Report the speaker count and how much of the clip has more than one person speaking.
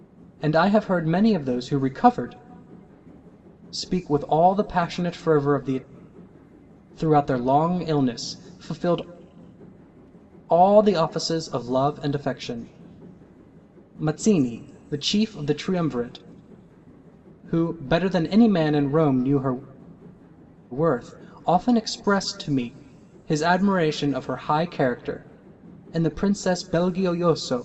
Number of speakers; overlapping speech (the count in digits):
1, no overlap